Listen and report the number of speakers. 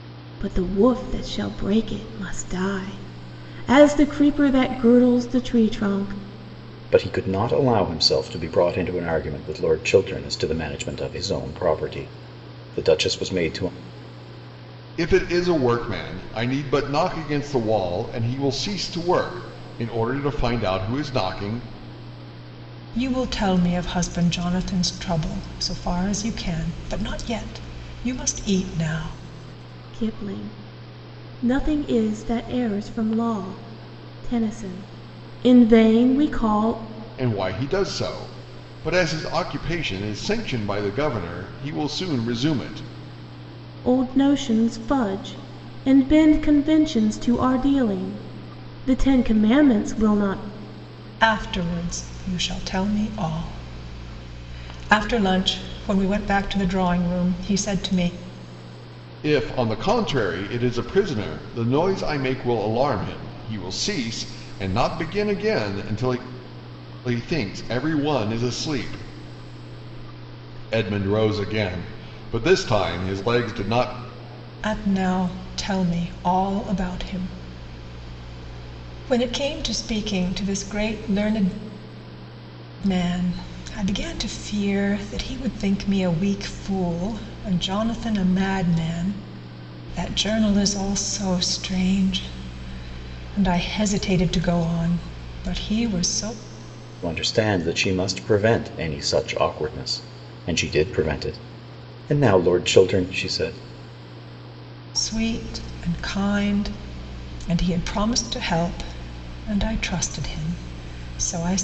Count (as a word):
four